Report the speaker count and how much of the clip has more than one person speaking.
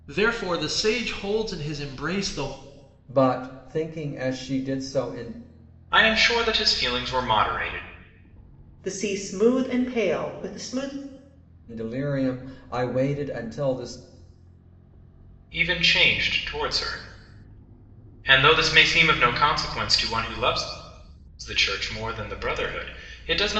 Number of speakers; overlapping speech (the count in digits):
4, no overlap